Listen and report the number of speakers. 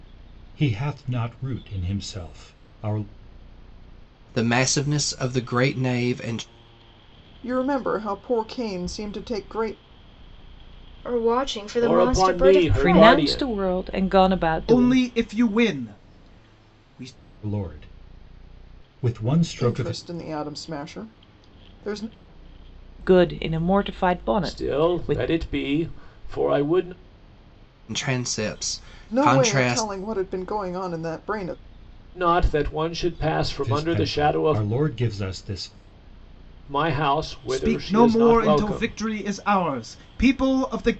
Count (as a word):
seven